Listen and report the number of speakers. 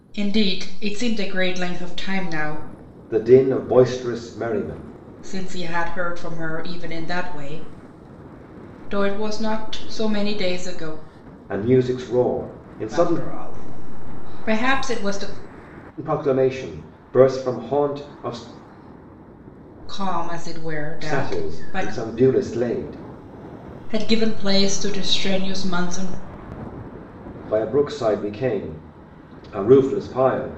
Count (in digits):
2